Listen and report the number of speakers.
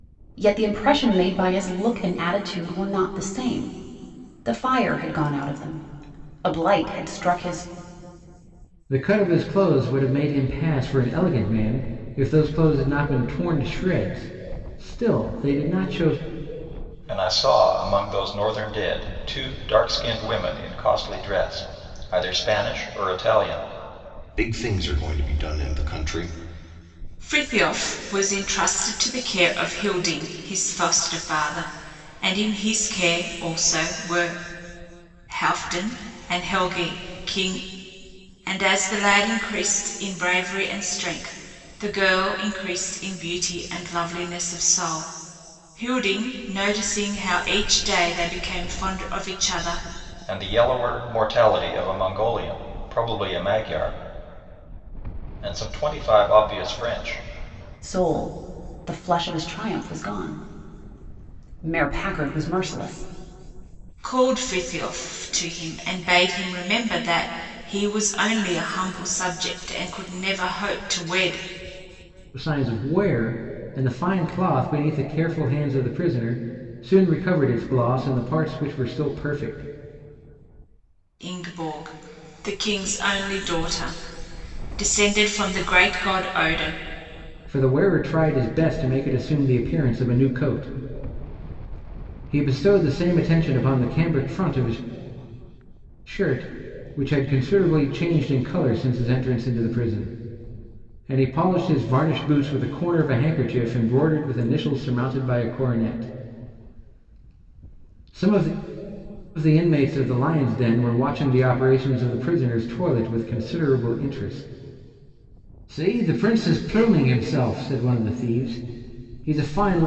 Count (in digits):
5